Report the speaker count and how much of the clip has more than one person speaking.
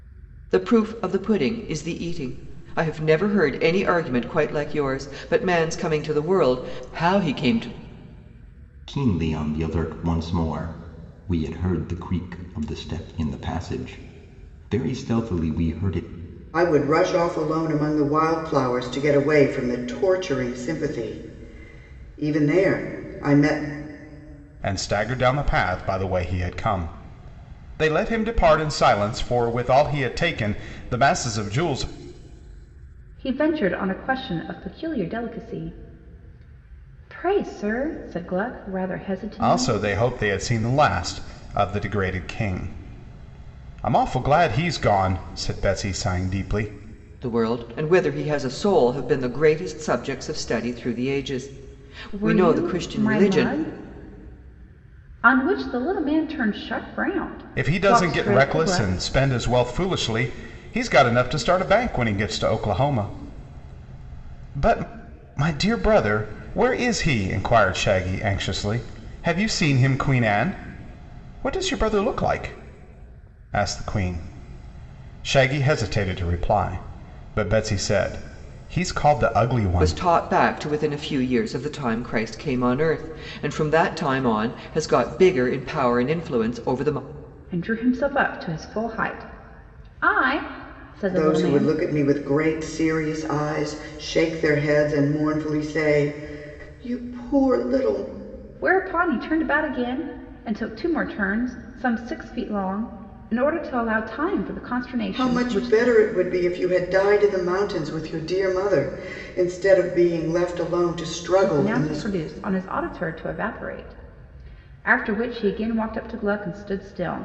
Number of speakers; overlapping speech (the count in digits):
5, about 5%